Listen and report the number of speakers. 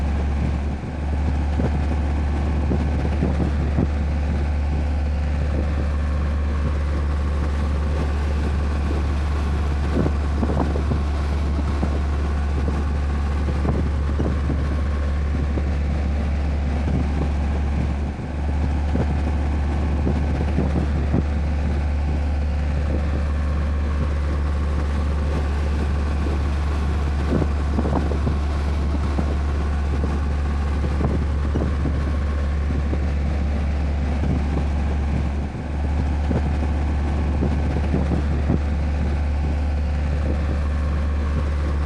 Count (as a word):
zero